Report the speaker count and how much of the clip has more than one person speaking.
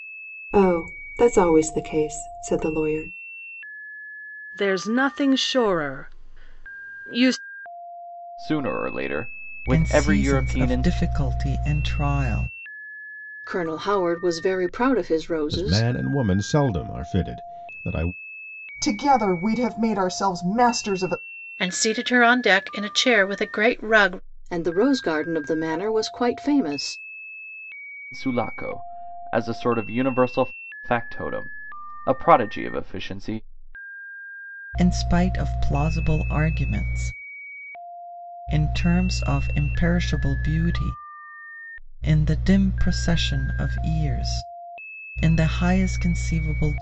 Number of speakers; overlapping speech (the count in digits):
8, about 3%